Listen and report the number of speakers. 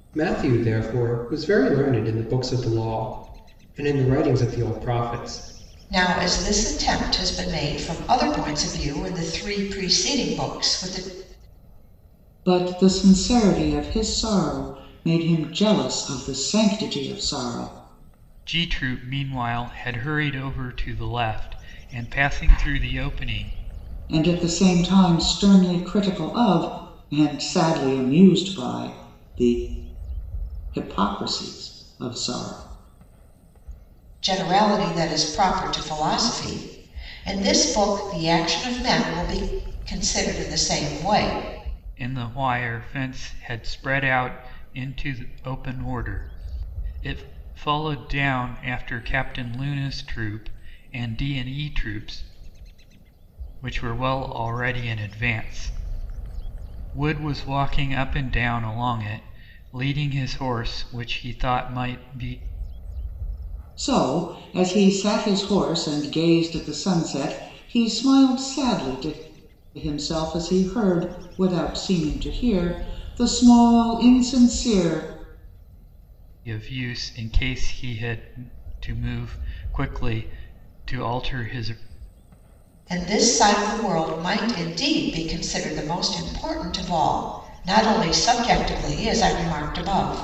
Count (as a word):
four